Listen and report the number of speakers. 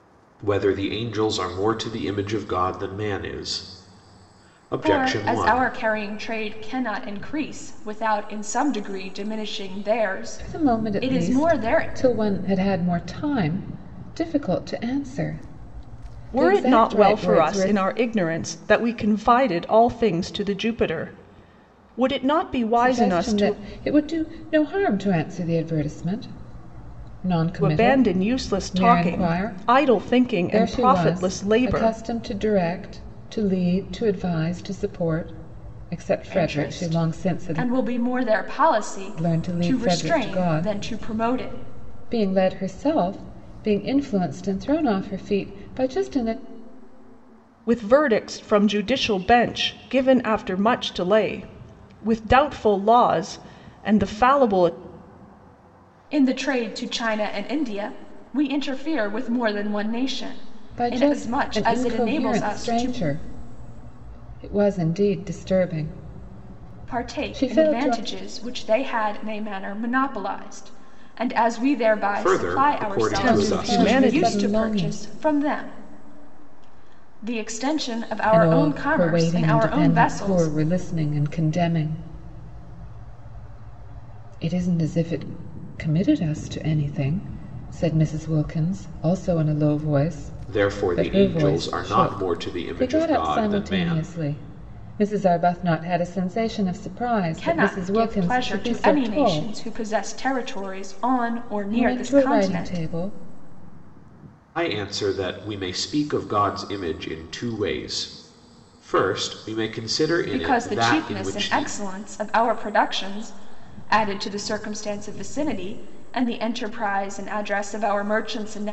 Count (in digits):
4